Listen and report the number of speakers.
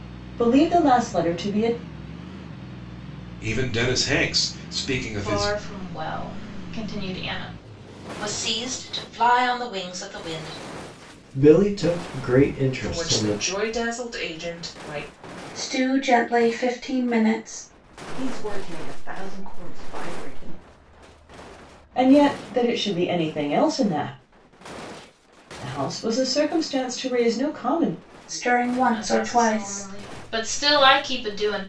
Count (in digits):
8